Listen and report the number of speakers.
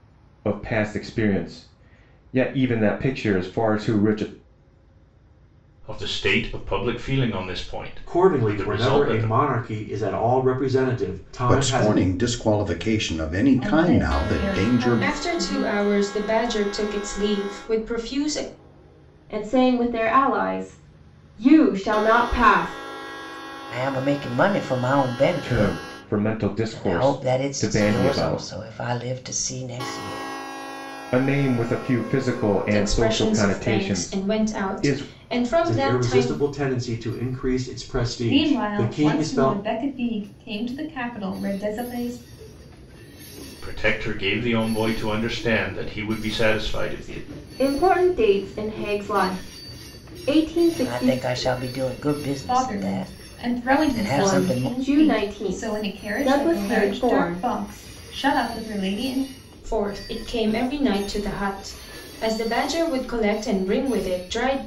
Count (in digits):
8